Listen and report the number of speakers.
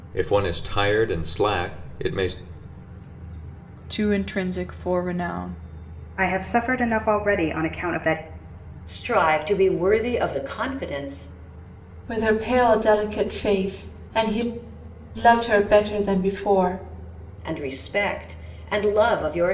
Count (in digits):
5